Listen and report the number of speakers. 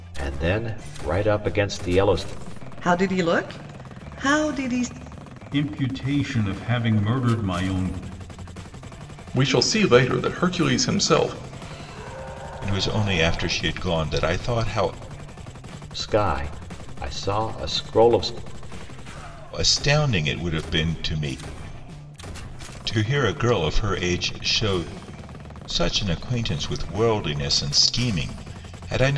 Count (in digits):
5